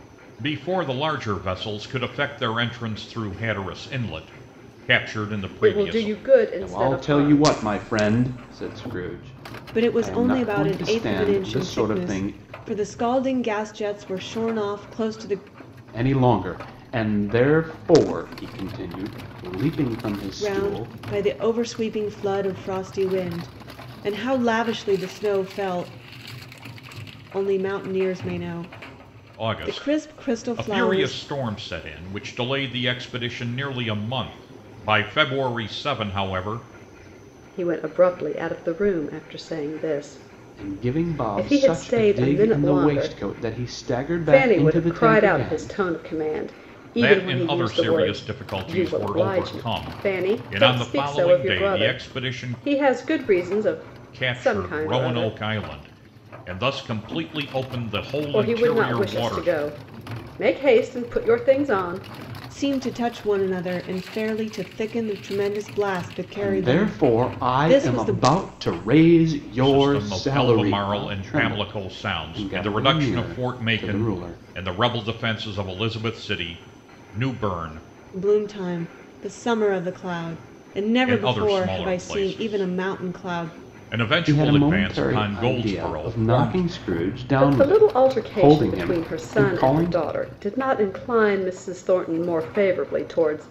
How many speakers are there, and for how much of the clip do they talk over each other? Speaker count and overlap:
four, about 35%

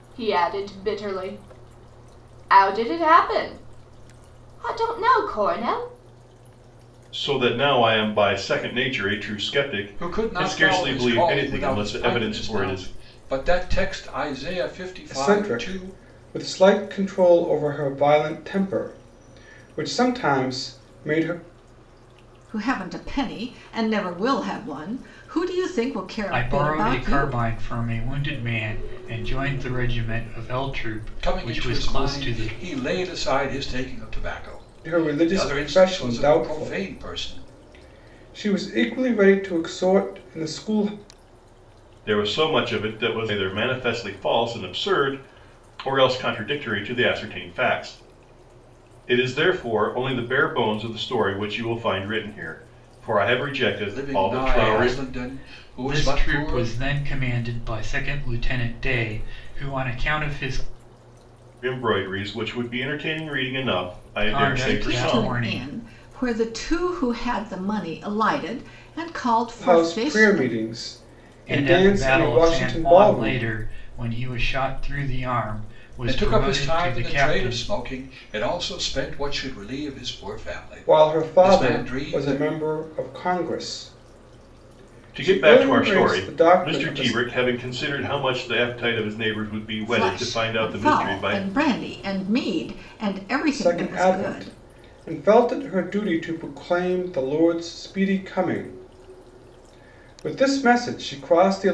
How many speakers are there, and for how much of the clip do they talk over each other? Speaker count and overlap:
six, about 24%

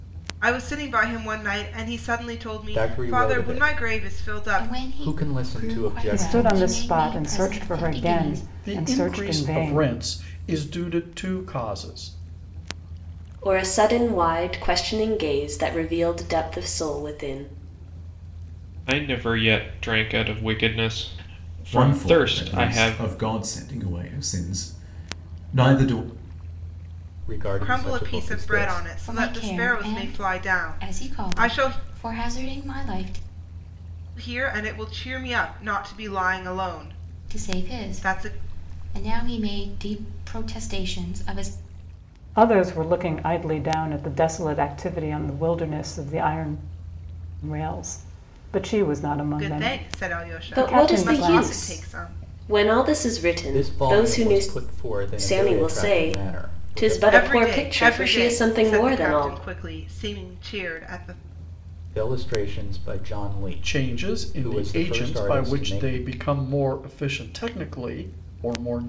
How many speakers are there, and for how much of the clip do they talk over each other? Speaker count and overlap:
eight, about 35%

